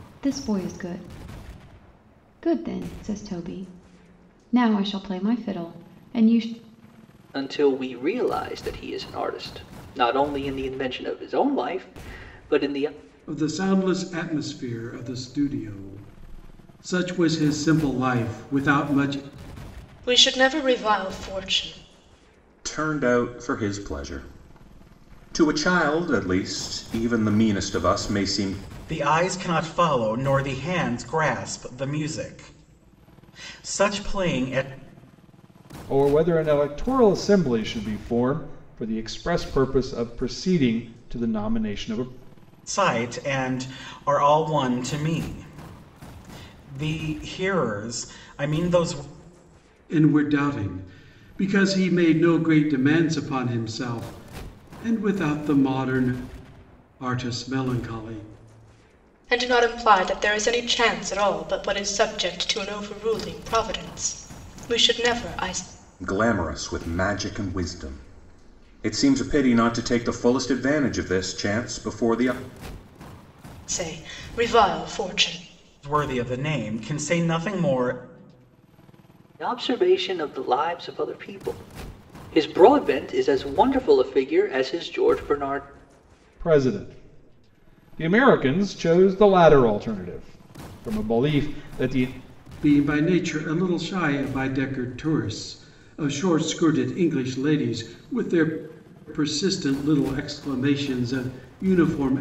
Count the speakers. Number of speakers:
7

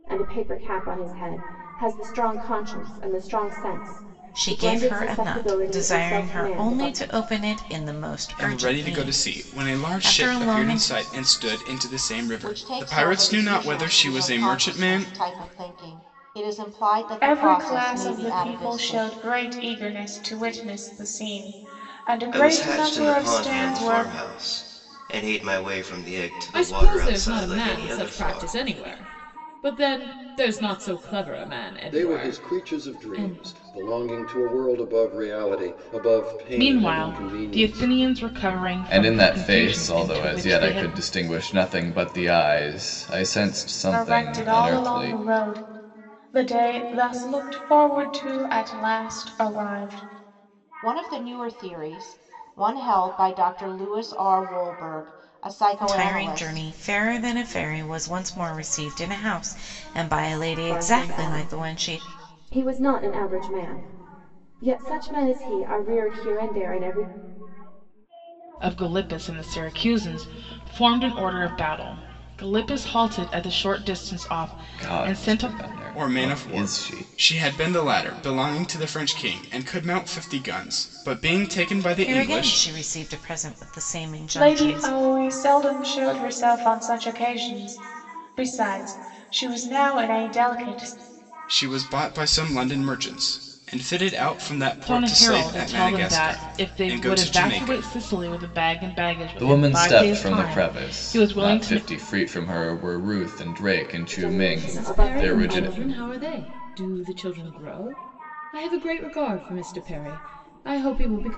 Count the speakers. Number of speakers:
10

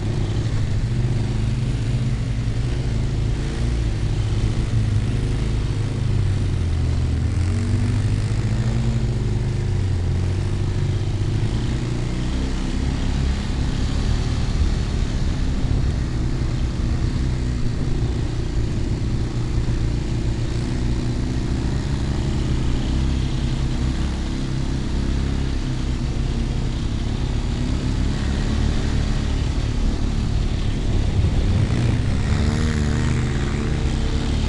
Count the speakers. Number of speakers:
0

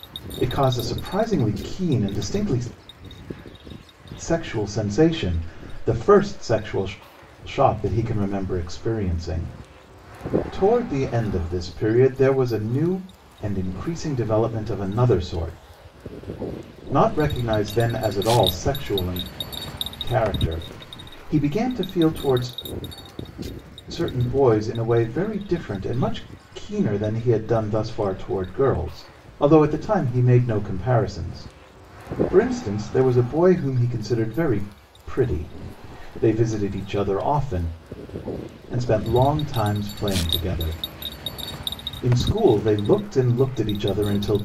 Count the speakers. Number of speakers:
1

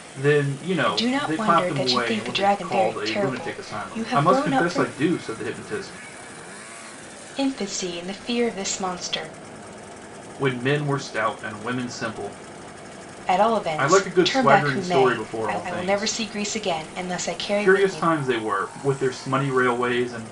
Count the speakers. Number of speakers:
2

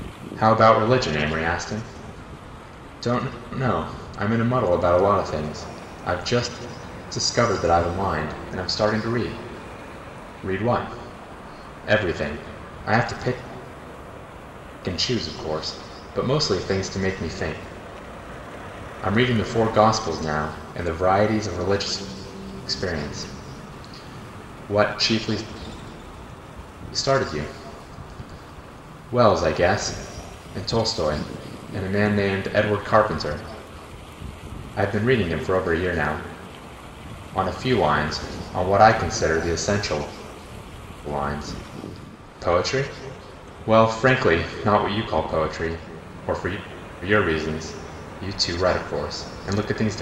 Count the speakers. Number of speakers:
1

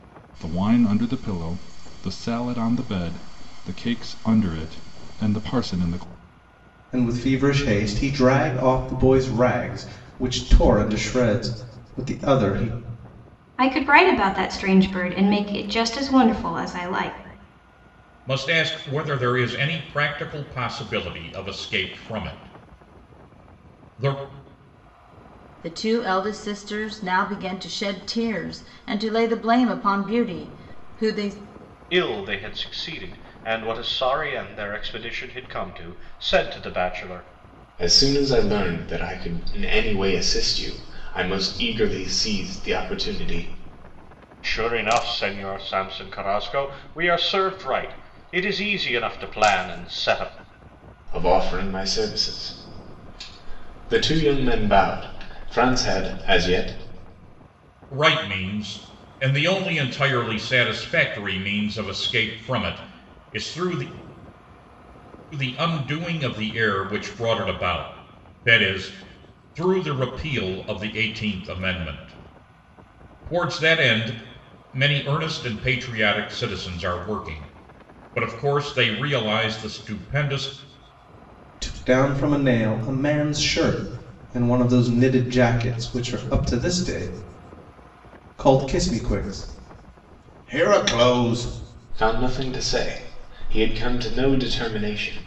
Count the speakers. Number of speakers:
7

